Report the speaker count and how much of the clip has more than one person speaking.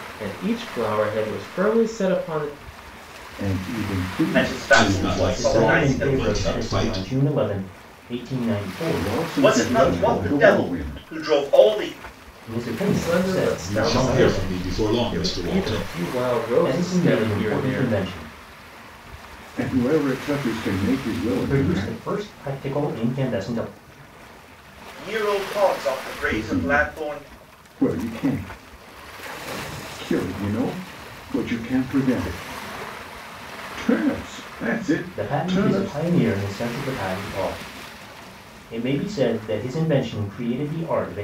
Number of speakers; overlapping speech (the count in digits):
5, about 29%